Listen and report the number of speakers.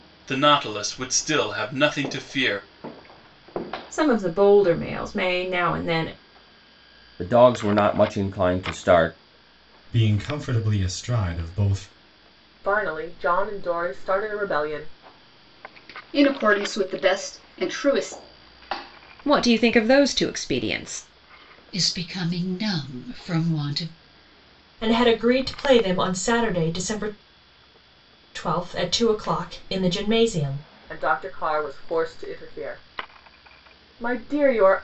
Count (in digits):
9